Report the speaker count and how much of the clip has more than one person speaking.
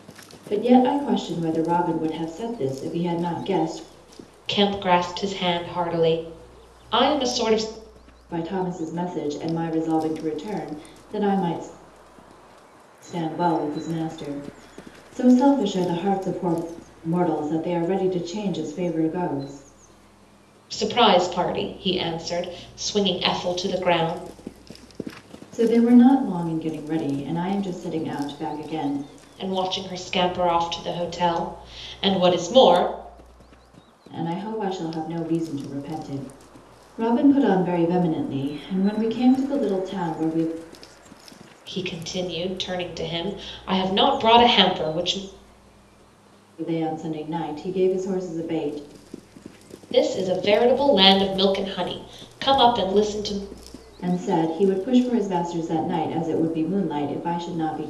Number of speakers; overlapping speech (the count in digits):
2, no overlap